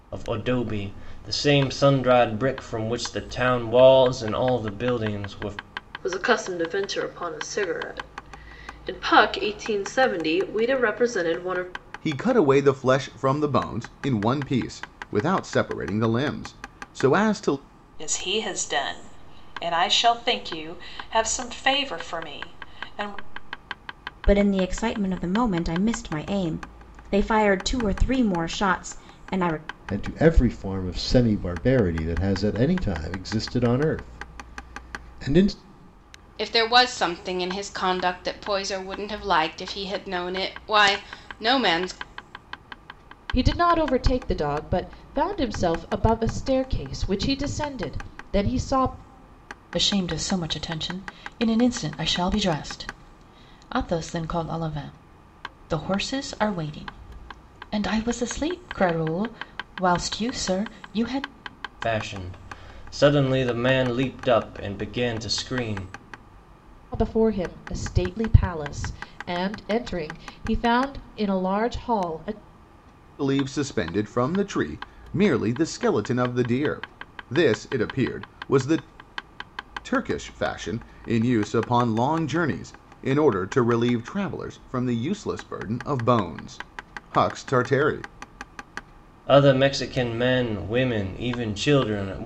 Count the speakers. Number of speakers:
9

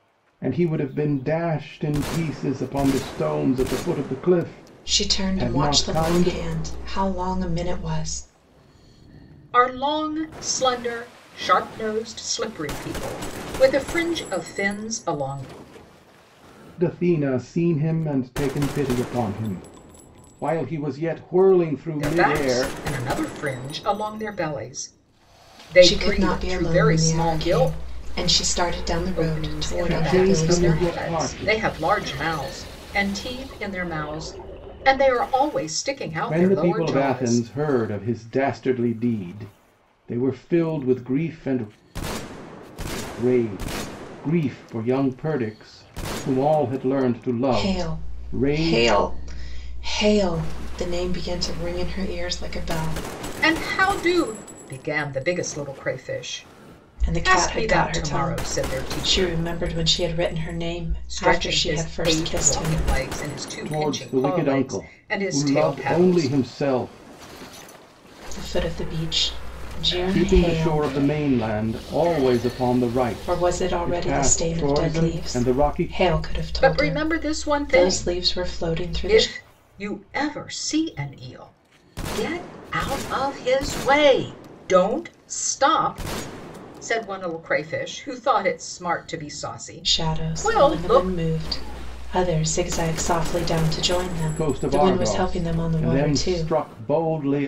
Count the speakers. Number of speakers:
3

